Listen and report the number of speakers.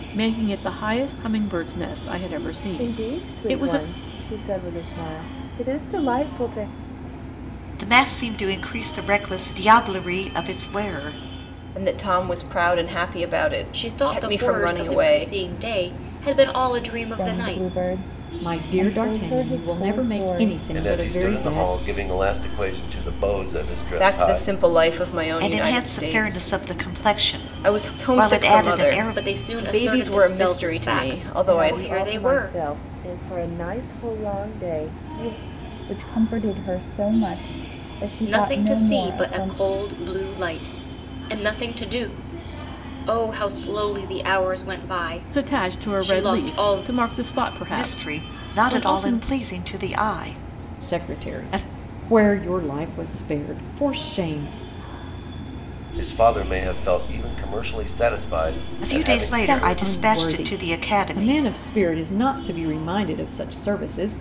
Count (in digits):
8